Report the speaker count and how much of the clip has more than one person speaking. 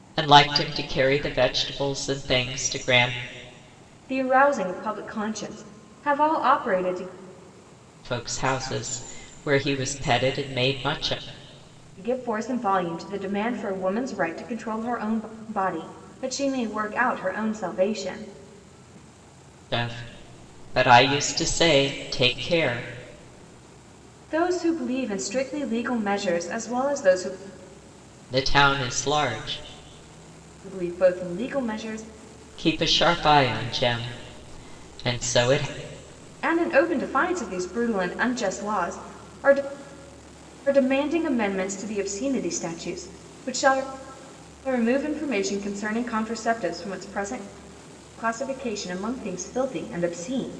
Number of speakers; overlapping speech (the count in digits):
2, no overlap